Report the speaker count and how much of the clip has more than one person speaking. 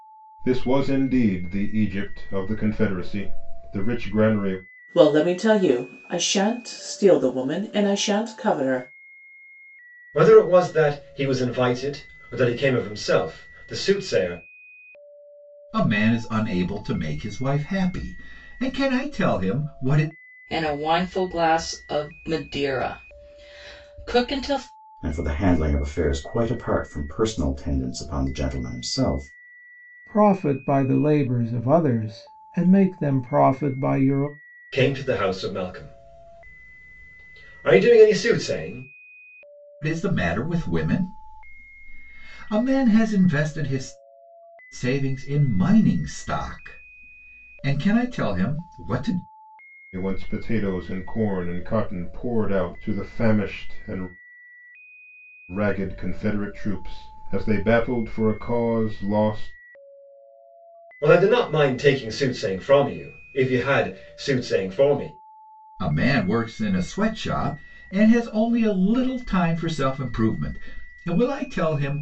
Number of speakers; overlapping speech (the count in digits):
7, no overlap